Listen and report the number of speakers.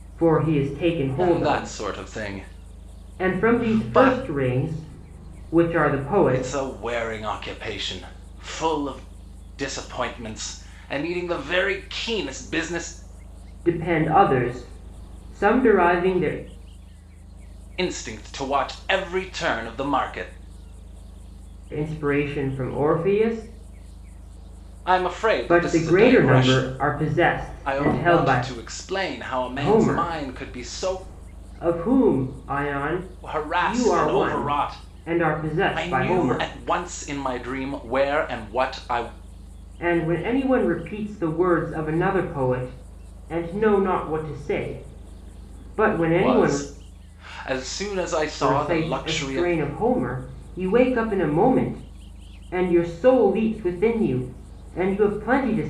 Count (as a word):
two